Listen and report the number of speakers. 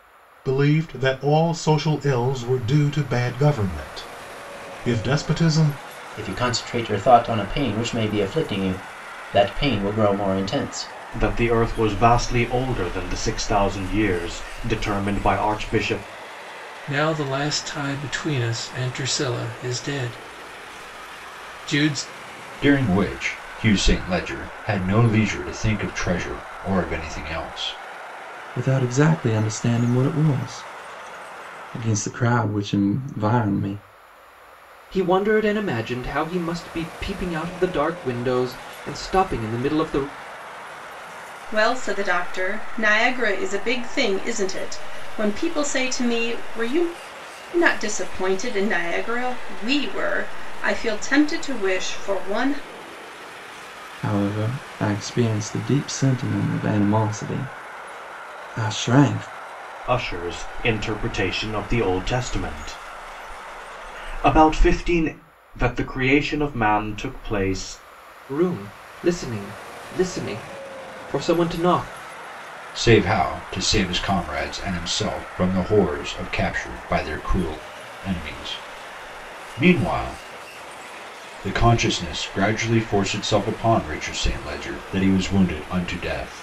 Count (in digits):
8